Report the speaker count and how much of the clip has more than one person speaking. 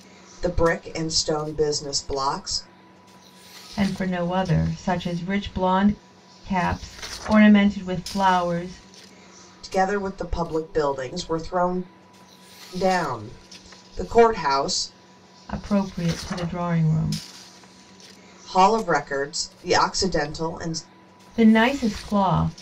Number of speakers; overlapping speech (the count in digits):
2, no overlap